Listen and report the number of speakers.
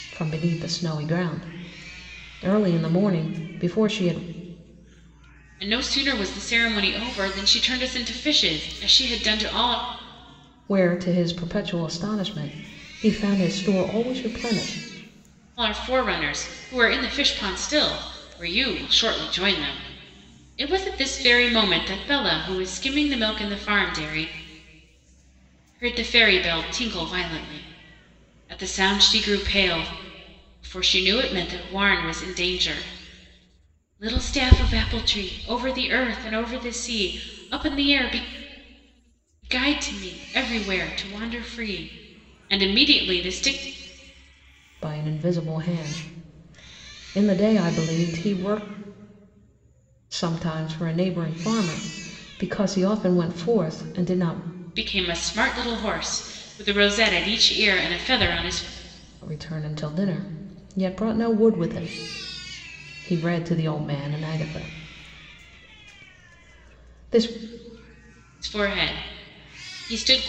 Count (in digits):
2